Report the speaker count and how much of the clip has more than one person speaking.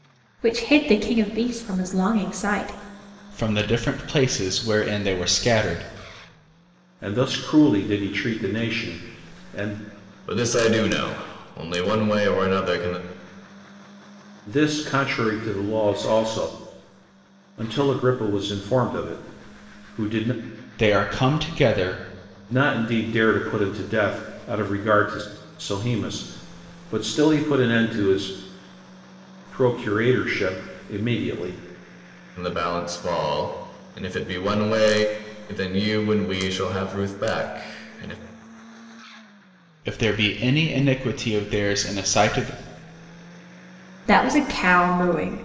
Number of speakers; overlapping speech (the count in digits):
4, no overlap